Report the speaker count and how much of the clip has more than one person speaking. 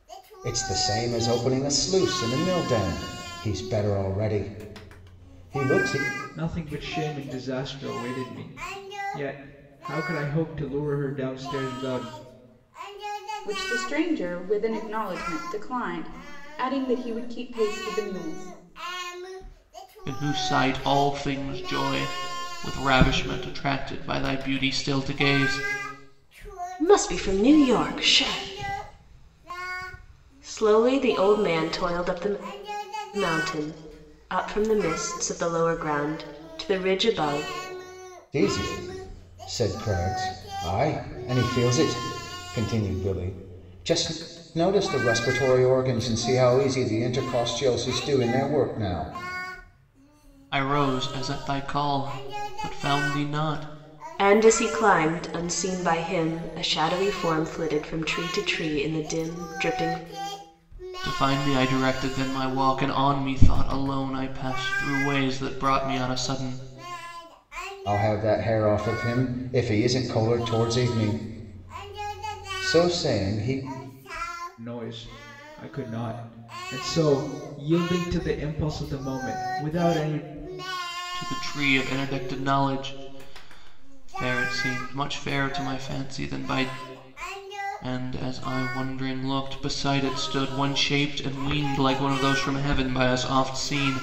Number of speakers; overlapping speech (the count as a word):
five, no overlap